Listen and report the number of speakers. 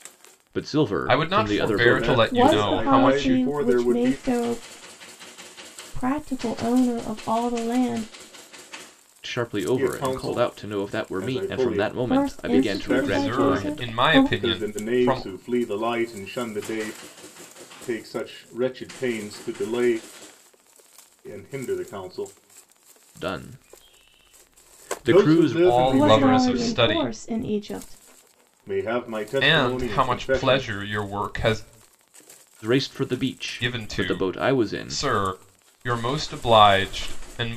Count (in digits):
4